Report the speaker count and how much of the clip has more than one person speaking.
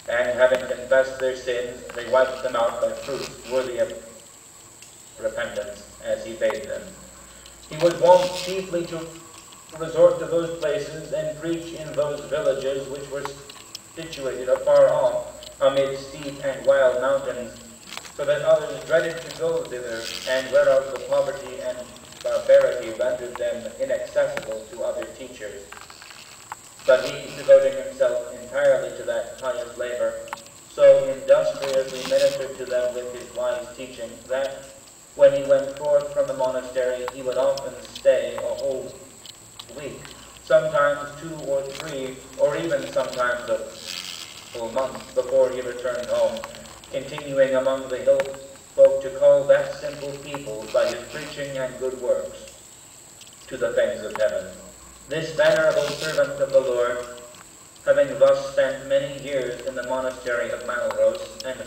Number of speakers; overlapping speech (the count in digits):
1, no overlap